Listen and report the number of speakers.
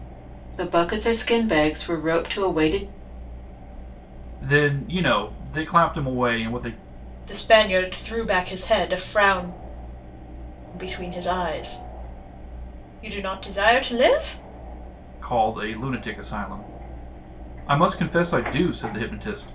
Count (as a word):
three